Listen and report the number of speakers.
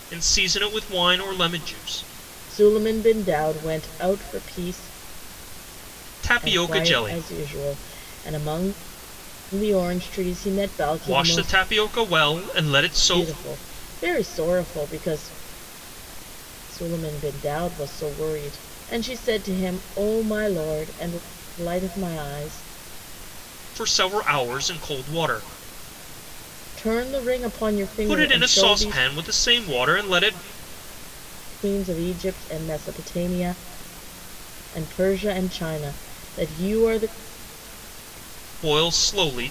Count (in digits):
2